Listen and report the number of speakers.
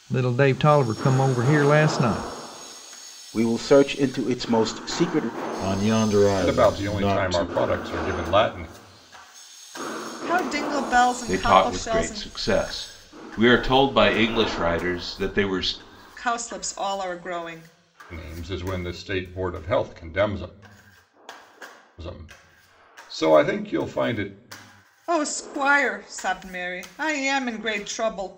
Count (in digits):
6